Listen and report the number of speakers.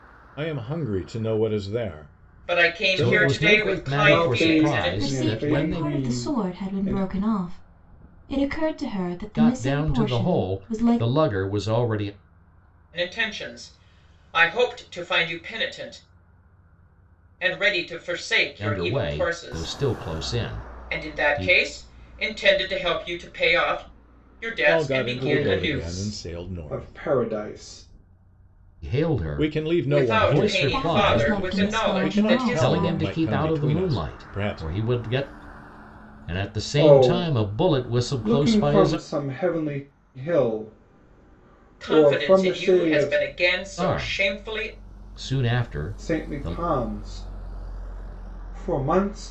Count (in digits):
5